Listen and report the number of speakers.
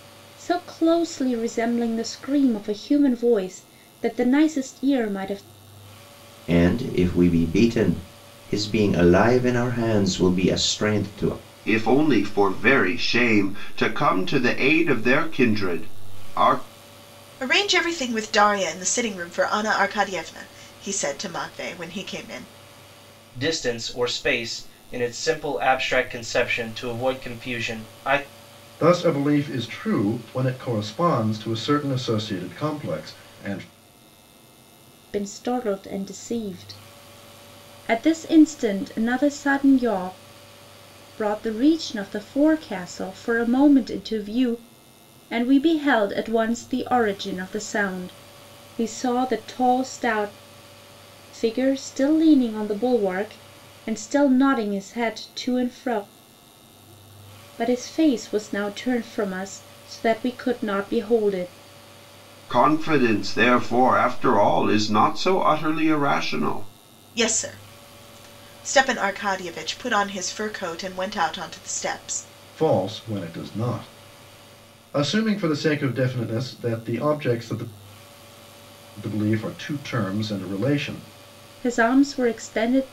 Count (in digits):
6